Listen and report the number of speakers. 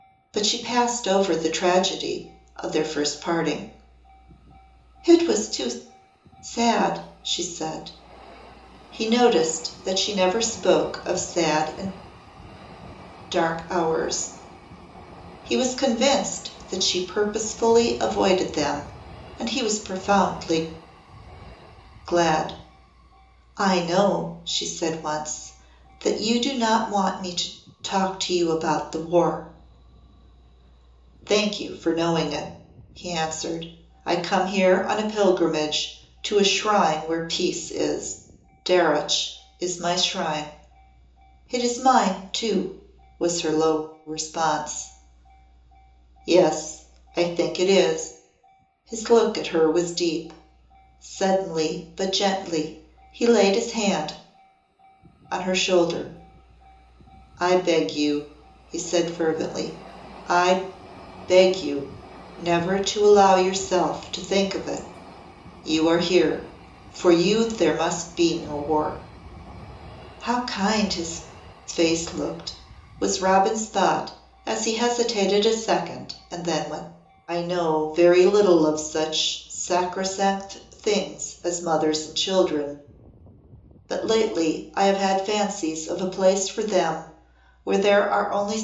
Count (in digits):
1